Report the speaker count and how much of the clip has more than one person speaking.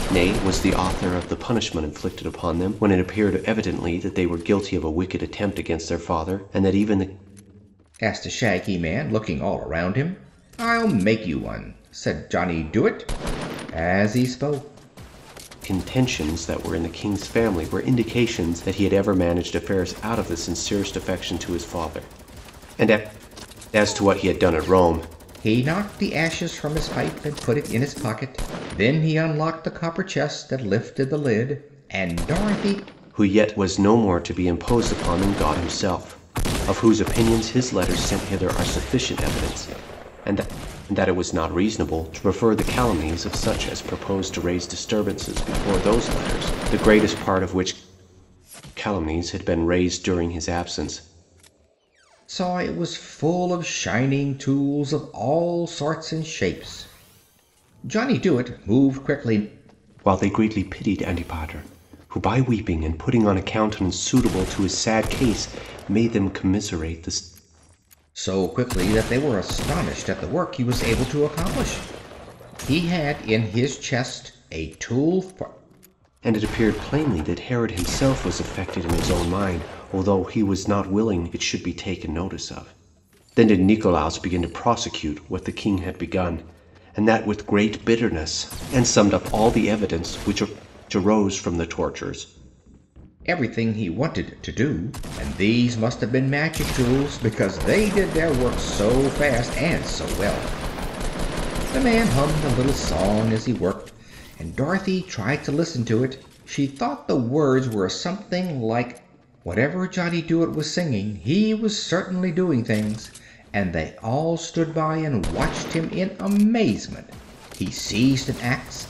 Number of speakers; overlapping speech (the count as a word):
two, no overlap